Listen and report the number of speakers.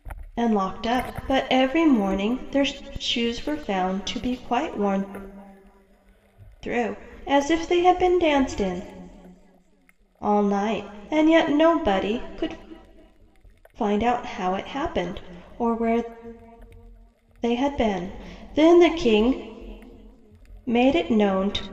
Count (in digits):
1